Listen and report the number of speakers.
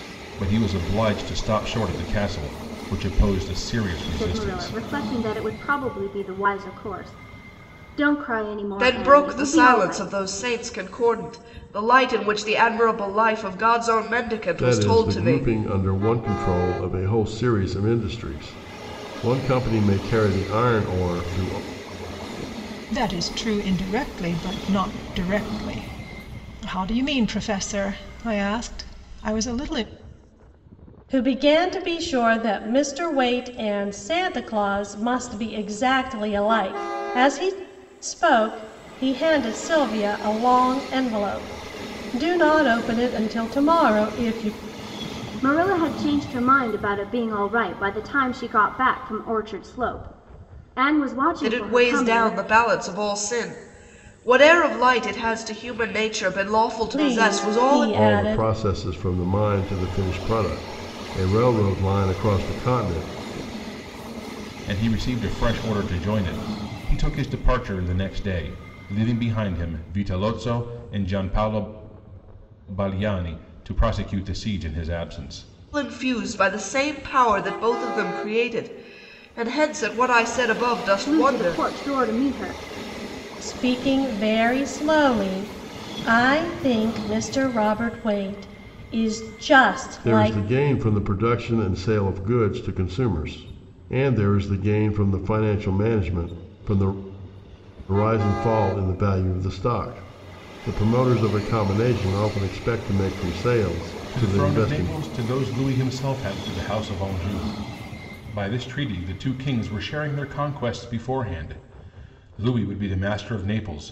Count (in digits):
6